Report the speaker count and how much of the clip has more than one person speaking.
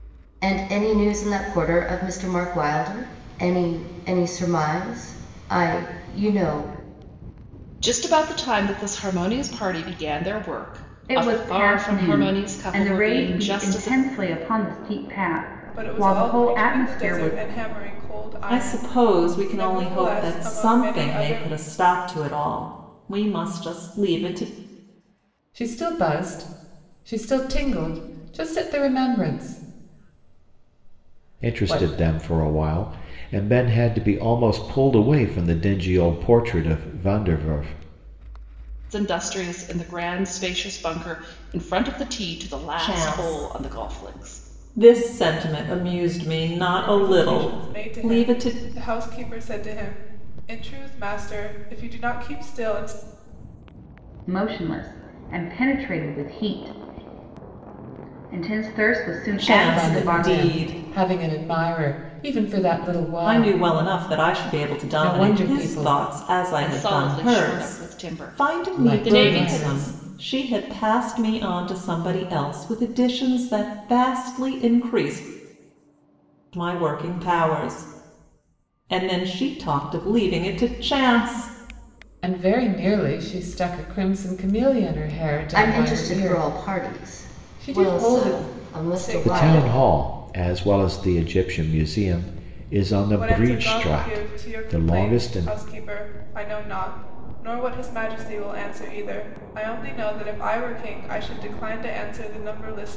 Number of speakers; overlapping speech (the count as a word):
seven, about 25%